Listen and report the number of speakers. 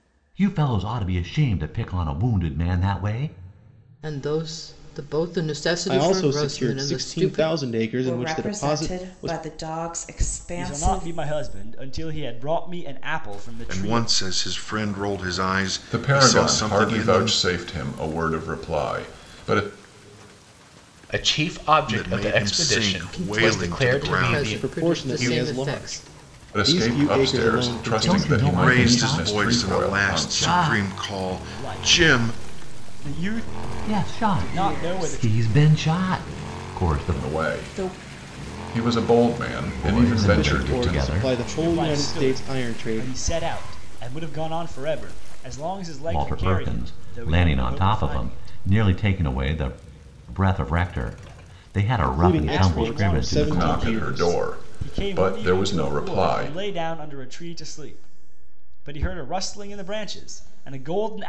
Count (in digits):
8